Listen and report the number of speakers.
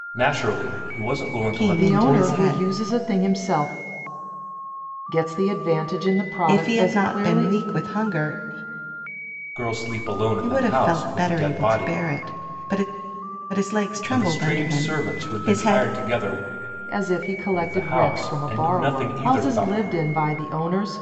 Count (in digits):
3